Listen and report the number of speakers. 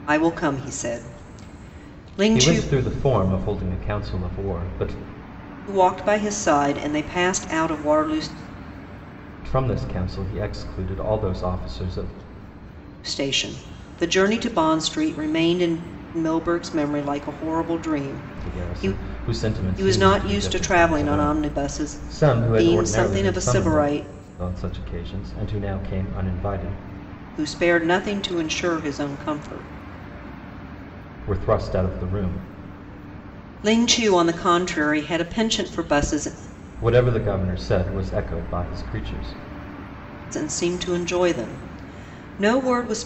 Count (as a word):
two